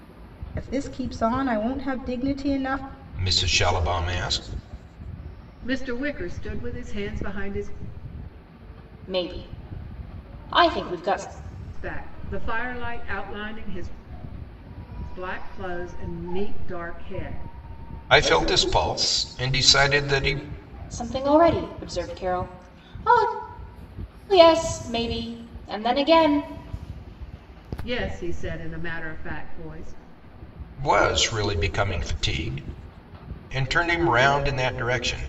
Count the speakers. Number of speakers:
four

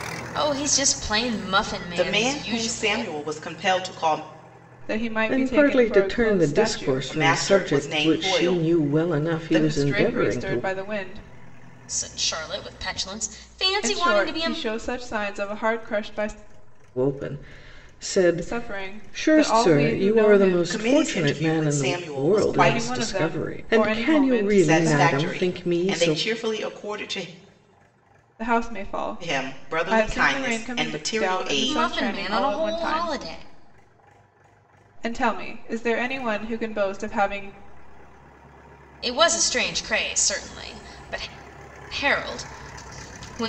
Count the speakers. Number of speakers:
four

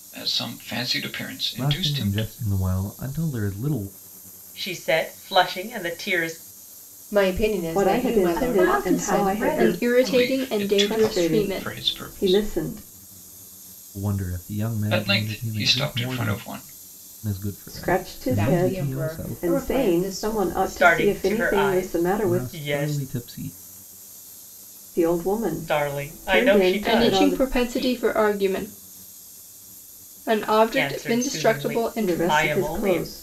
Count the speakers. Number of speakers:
seven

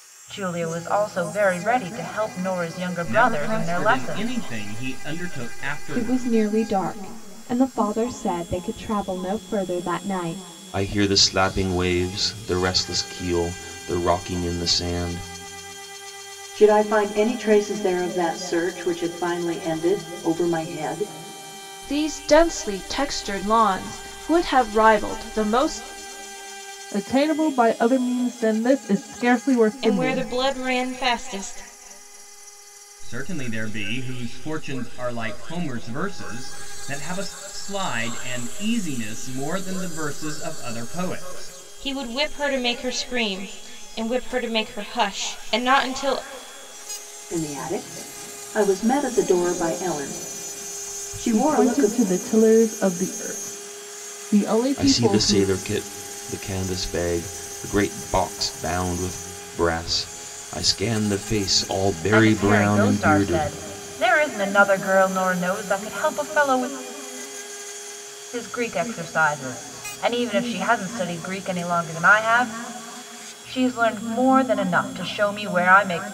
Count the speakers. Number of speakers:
eight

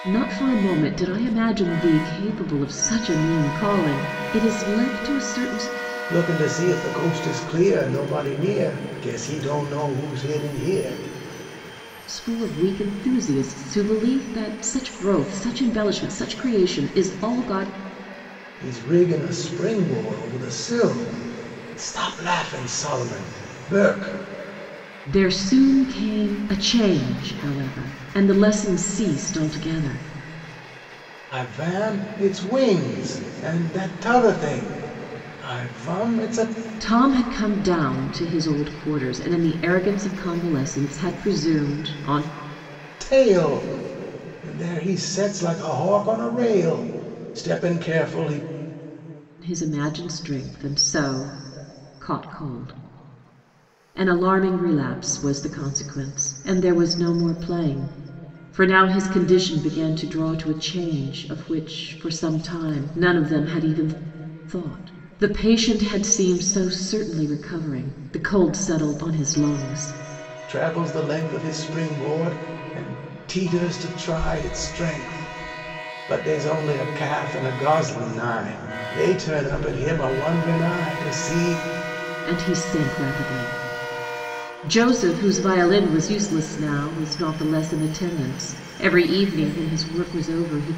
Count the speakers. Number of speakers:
two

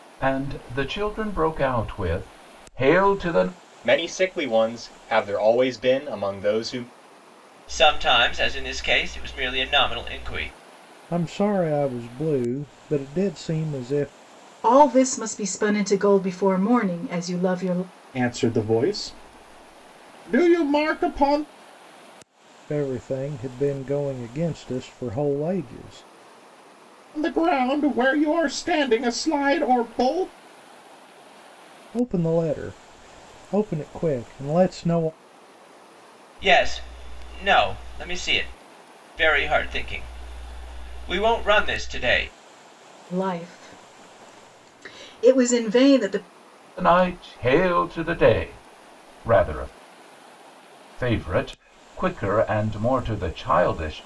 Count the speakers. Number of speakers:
six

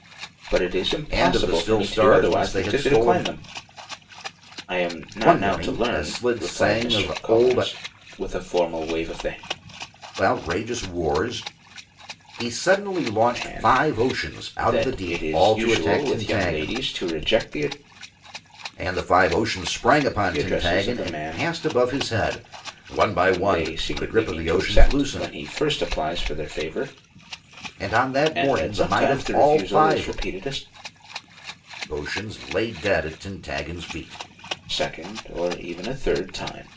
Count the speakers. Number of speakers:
two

